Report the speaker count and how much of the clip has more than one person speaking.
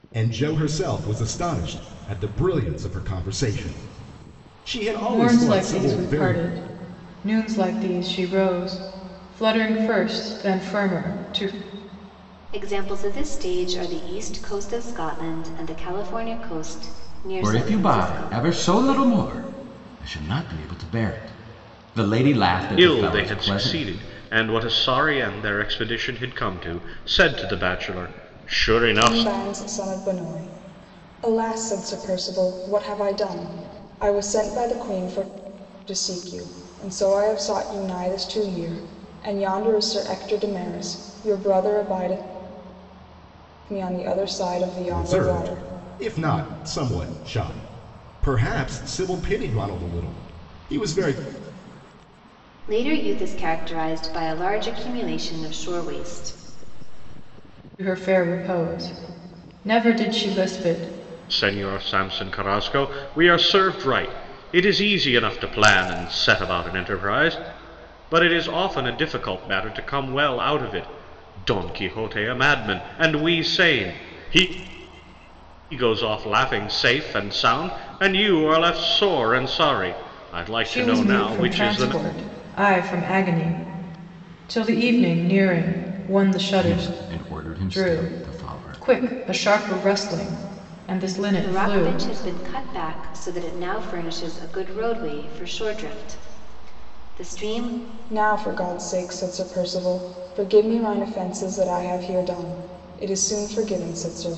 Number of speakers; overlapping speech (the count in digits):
6, about 8%